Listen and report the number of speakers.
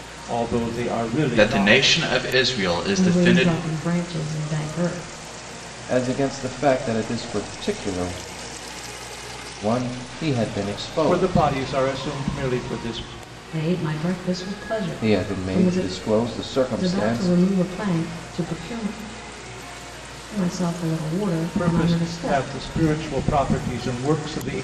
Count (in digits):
4